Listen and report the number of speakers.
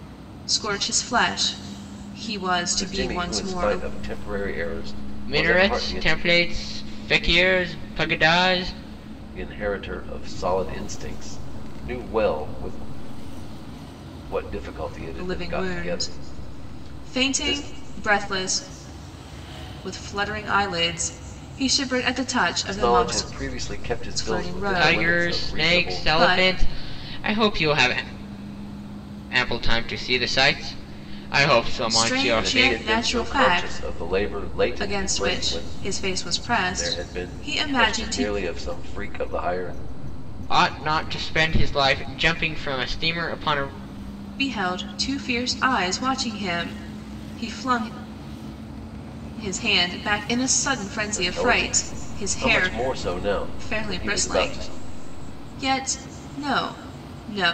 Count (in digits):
3